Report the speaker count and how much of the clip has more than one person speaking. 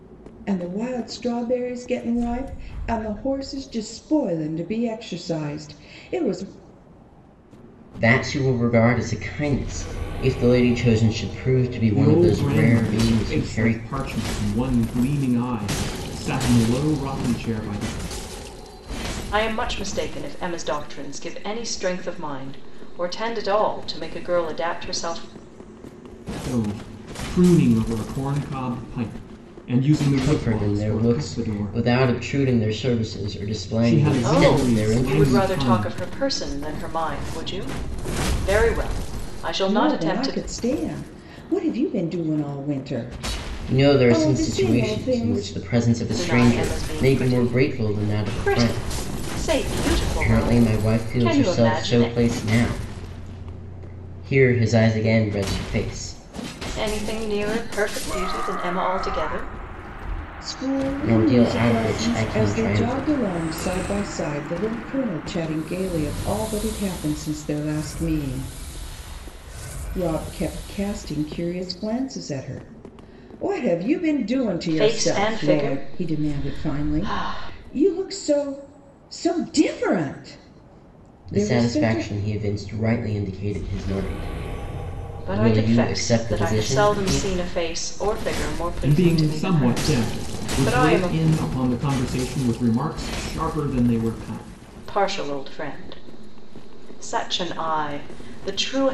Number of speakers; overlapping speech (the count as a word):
four, about 24%